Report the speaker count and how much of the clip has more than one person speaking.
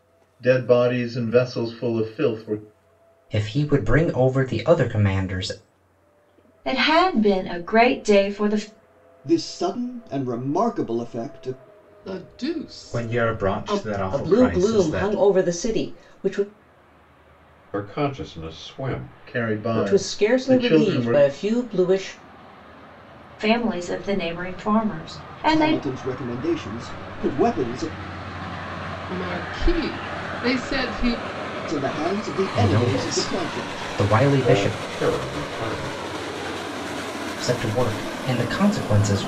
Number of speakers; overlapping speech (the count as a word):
eight, about 16%